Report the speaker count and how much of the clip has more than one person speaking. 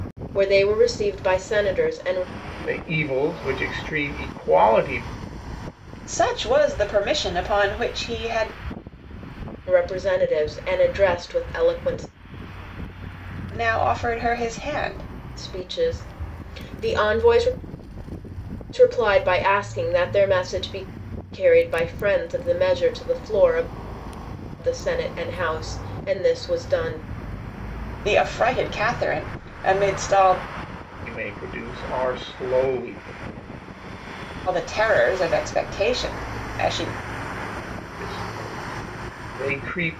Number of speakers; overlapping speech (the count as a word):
three, no overlap